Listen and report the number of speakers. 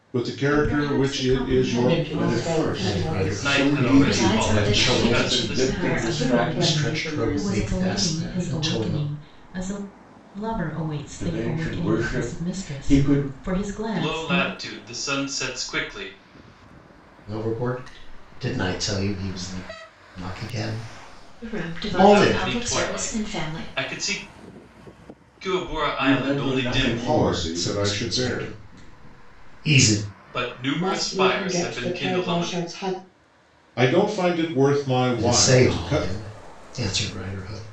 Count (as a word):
seven